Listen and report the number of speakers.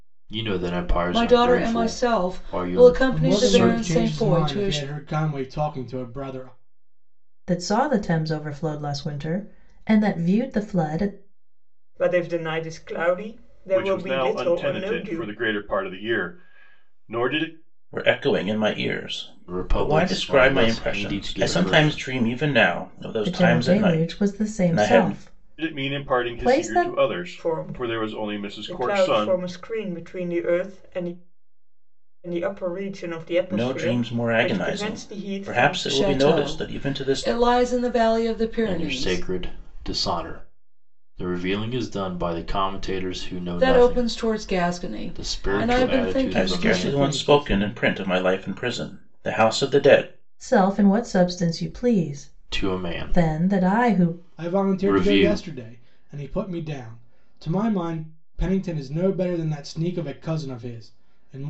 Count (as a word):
seven